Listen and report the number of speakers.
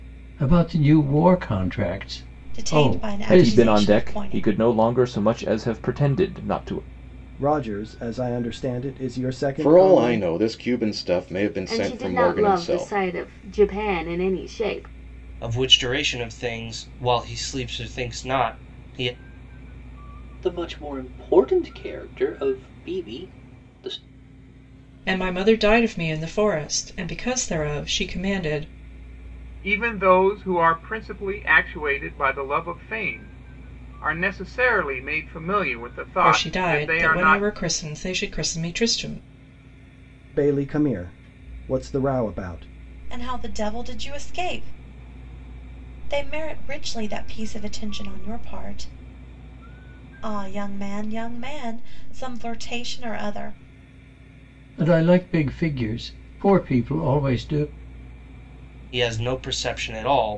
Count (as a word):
ten